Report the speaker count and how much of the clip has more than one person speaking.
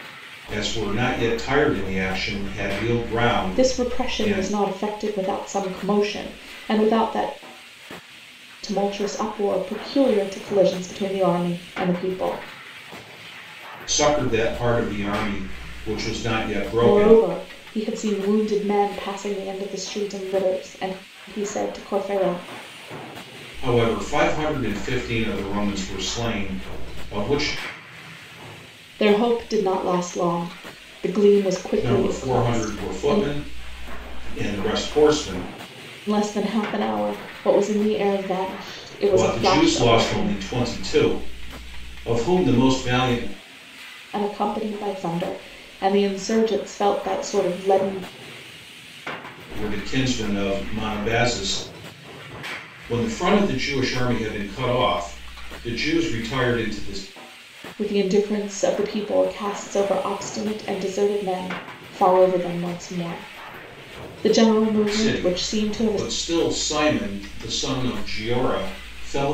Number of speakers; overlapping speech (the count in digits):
2, about 8%